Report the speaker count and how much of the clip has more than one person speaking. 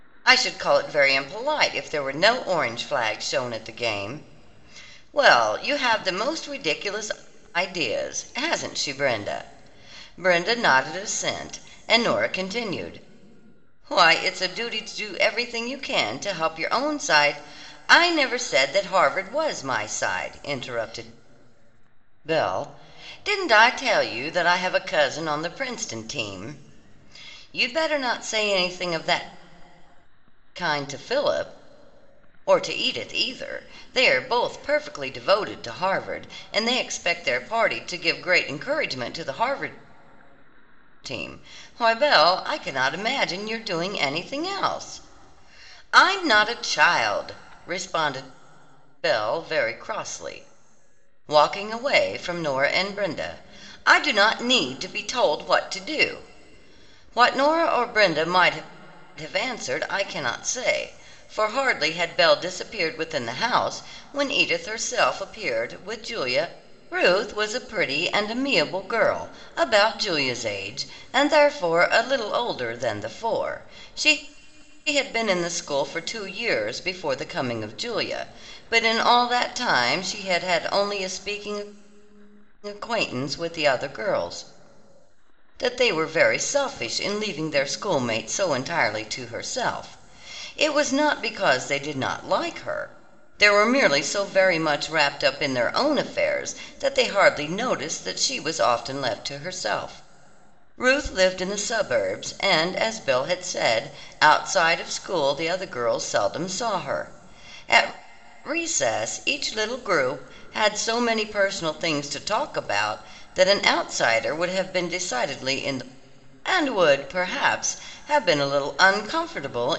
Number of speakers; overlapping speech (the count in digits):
1, no overlap